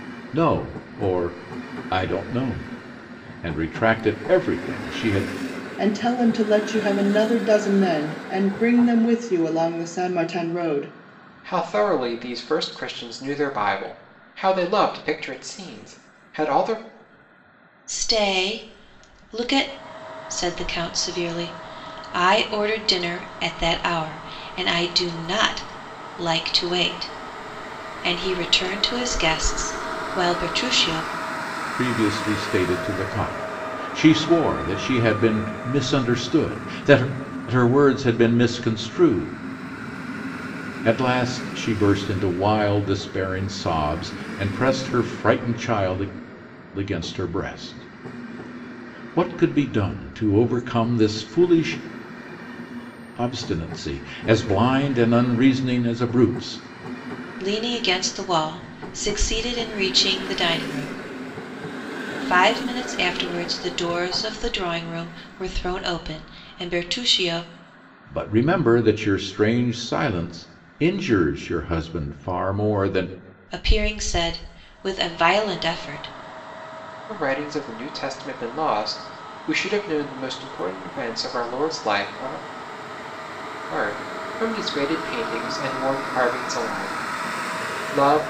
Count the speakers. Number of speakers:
4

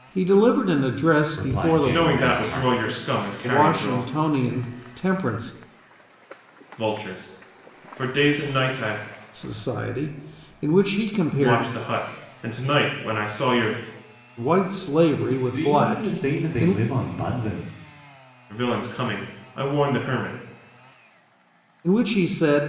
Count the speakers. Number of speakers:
3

